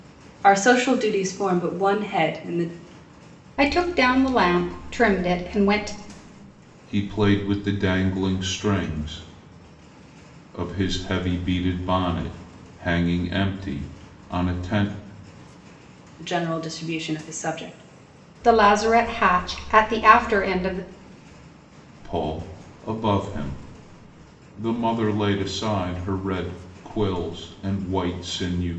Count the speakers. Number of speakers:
3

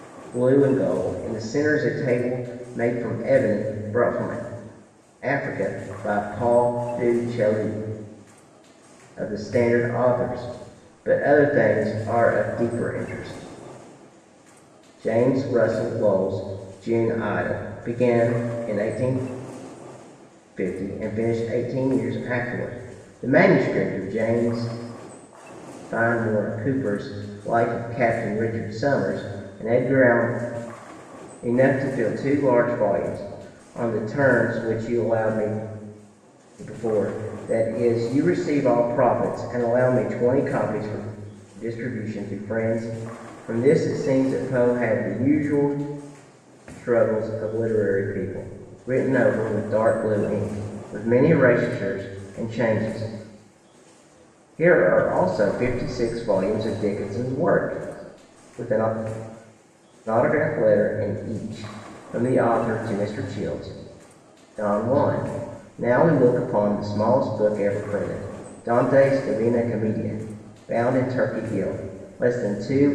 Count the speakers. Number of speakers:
1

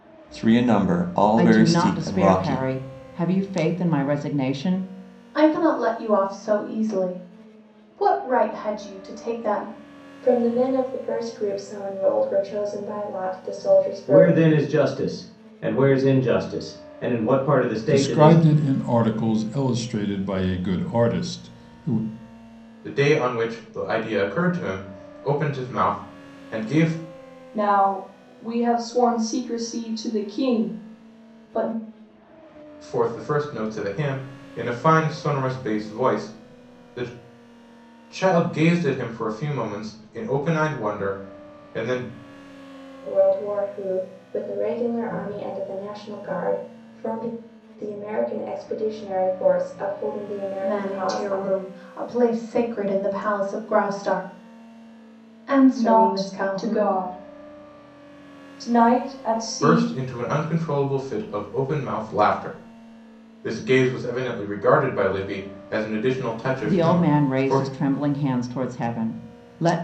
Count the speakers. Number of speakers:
8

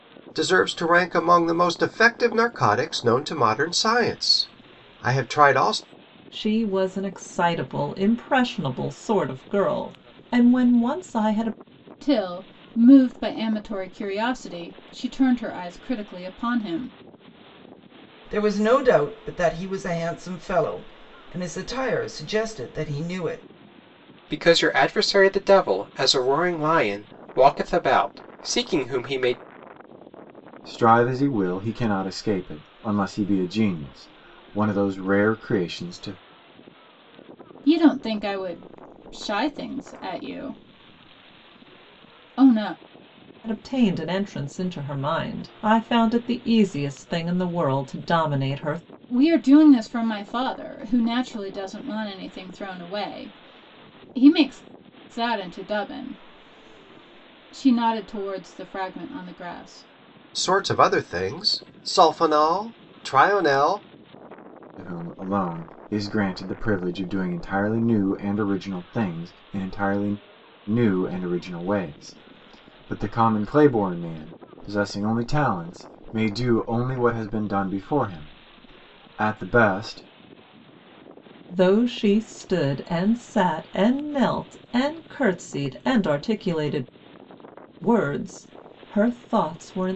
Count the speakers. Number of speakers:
6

